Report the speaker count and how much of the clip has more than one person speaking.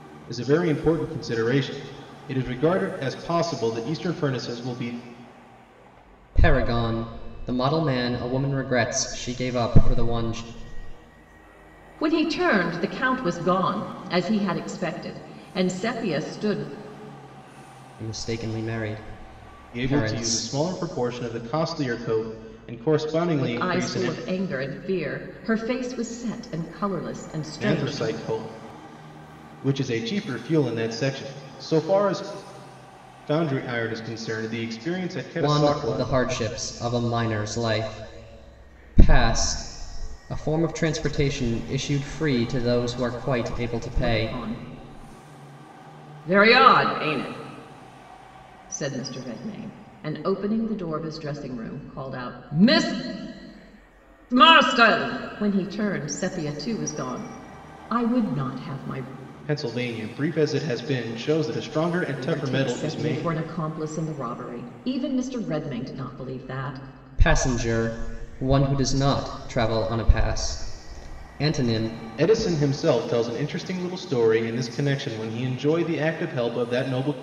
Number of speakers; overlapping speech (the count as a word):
three, about 6%